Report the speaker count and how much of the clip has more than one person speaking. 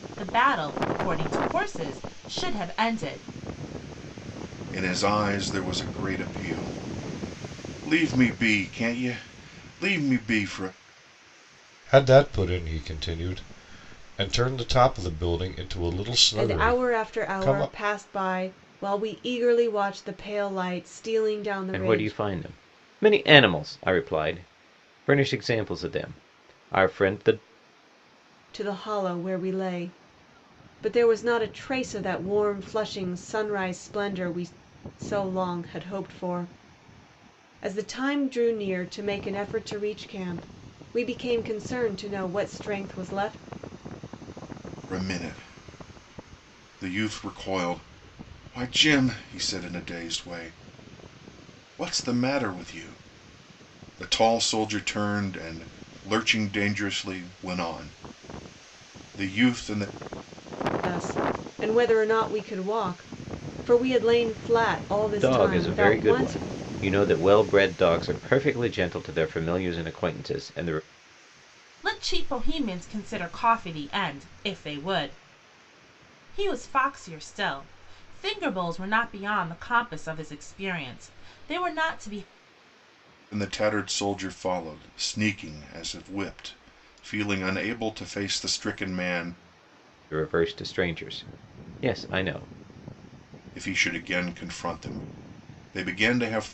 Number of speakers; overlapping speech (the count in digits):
5, about 3%